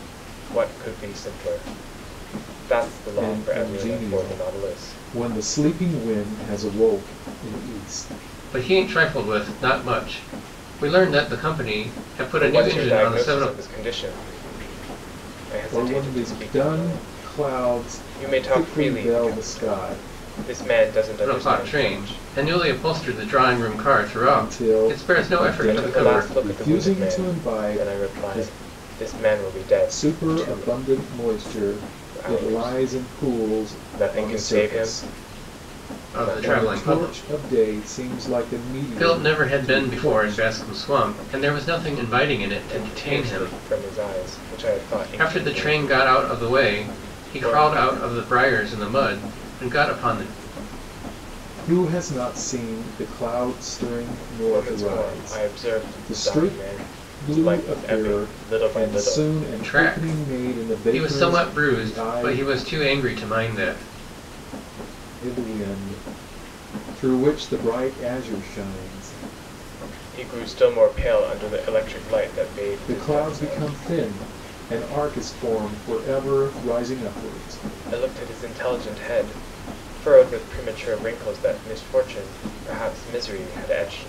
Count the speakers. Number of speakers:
three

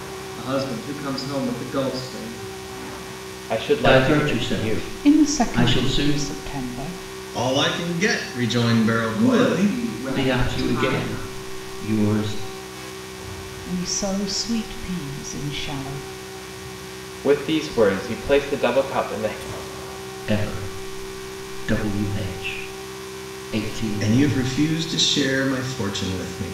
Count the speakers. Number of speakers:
five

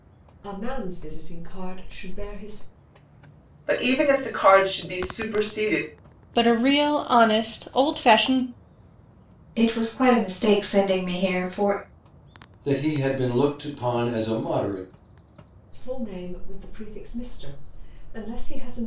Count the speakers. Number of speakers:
five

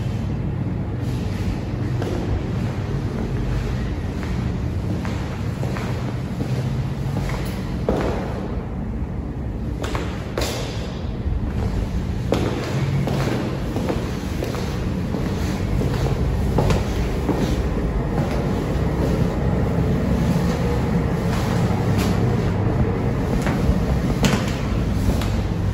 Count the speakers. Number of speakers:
zero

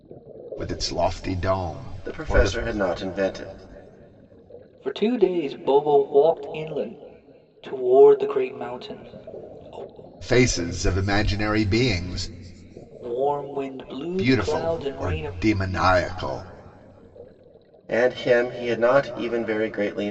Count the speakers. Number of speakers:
three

